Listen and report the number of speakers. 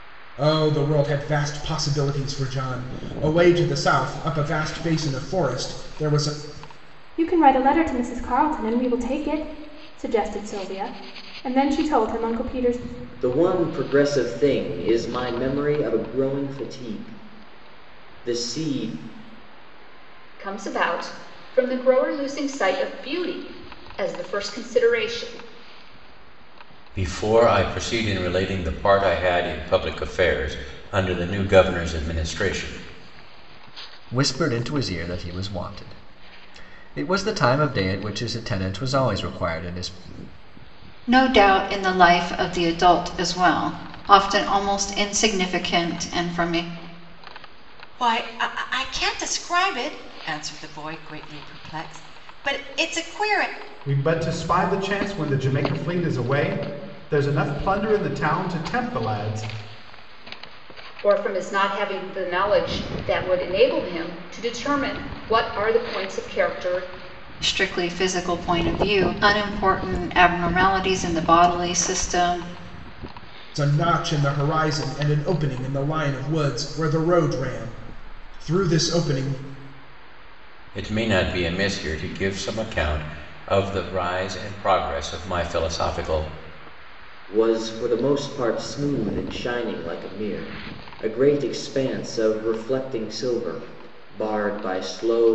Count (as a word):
nine